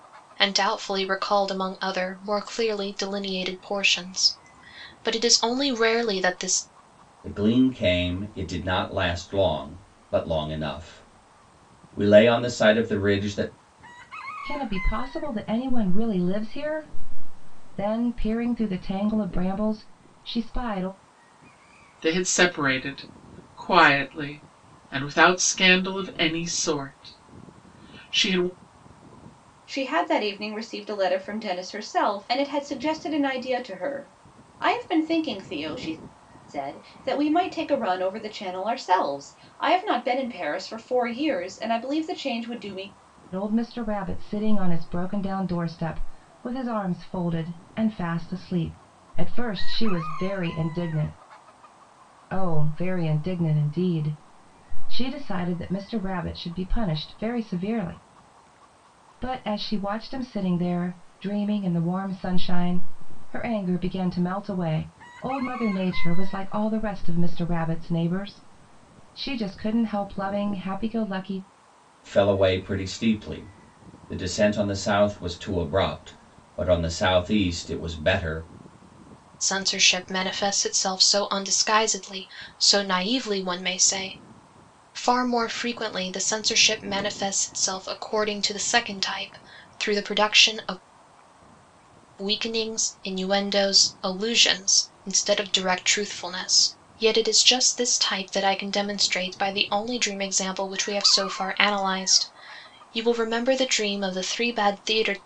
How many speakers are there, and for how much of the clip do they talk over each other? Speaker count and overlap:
five, no overlap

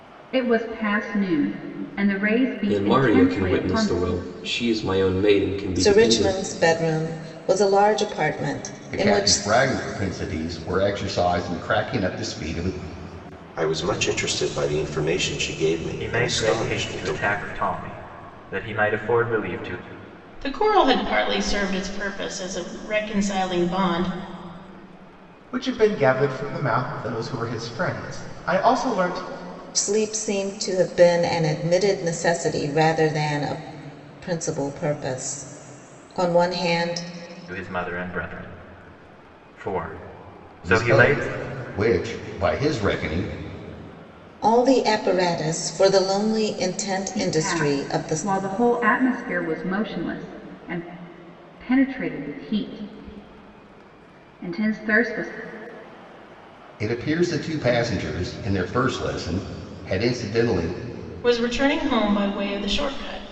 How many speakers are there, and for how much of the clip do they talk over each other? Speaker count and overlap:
eight, about 9%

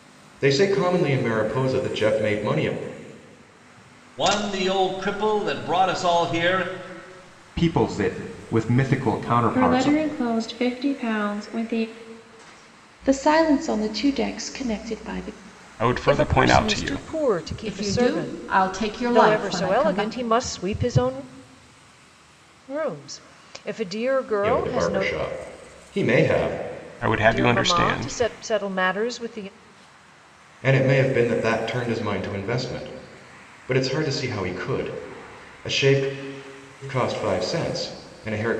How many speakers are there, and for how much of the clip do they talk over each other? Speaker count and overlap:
eight, about 13%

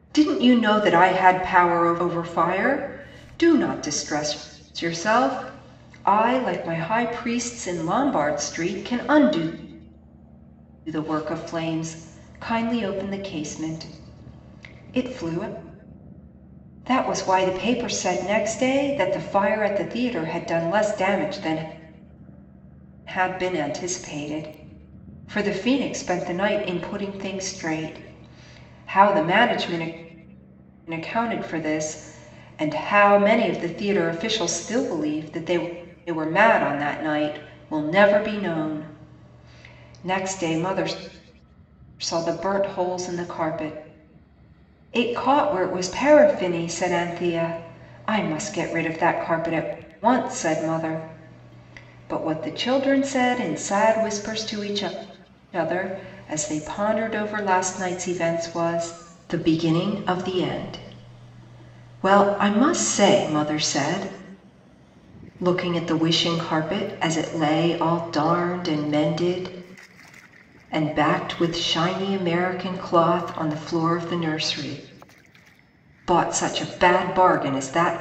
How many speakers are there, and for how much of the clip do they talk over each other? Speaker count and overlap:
one, no overlap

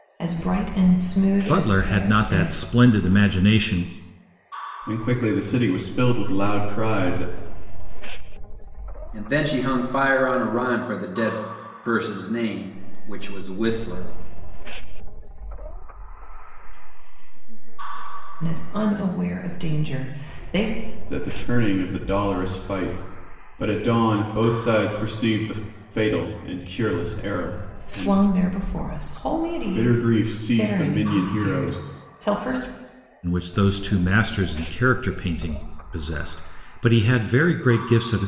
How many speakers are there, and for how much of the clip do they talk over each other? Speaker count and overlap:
five, about 22%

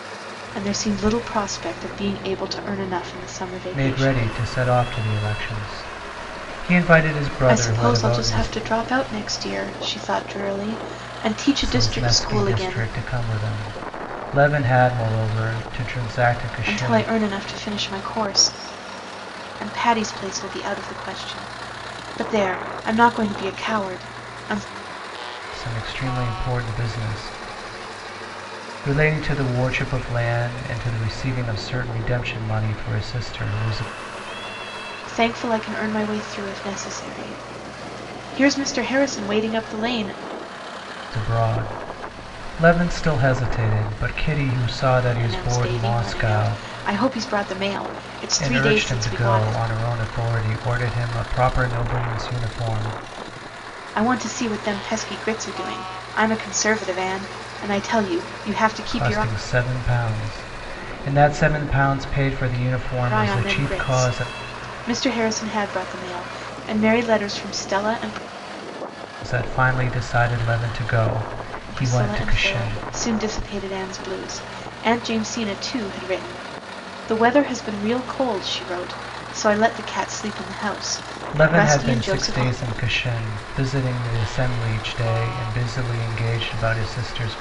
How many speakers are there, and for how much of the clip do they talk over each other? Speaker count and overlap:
two, about 11%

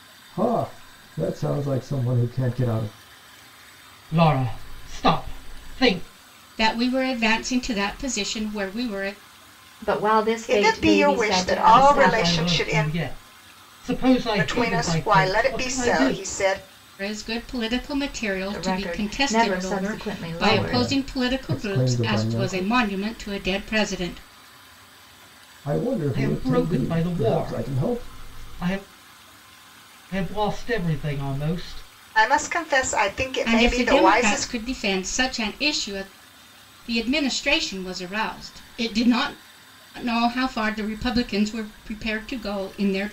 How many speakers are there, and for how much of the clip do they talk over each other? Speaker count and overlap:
five, about 27%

